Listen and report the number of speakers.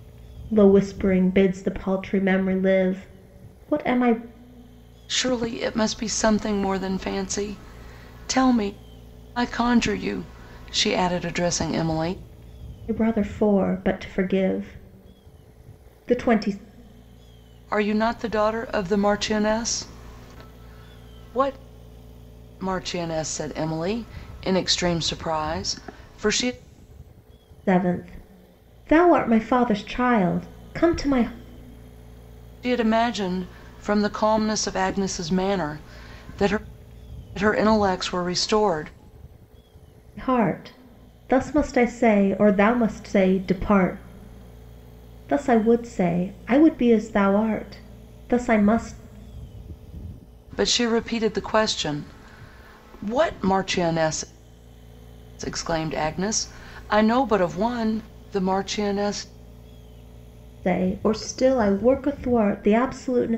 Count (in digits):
2